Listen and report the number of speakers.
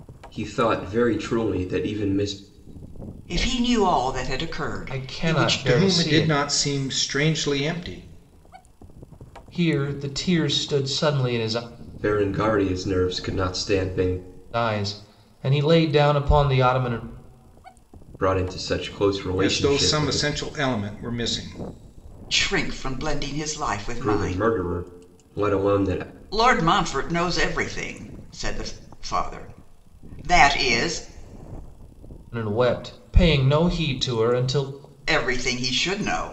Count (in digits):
4